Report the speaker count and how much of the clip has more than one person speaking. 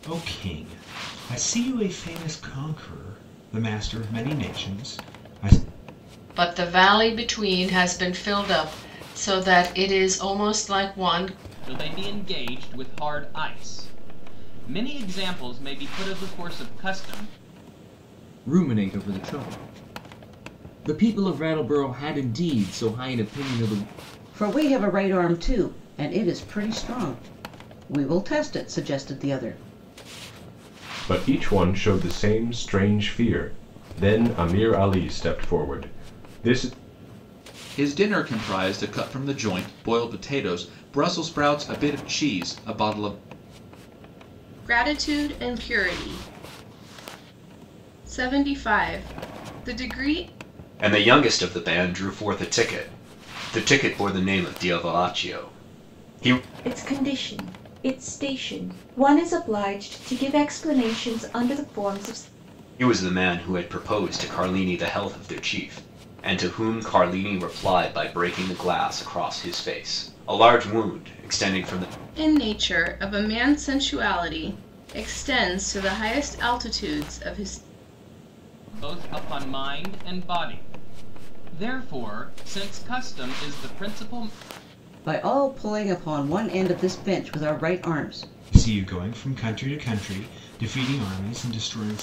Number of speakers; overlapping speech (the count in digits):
10, no overlap